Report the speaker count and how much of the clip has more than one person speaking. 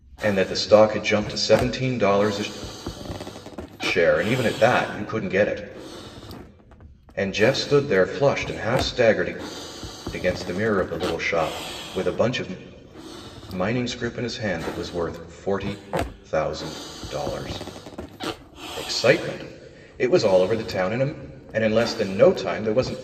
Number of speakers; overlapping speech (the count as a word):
one, no overlap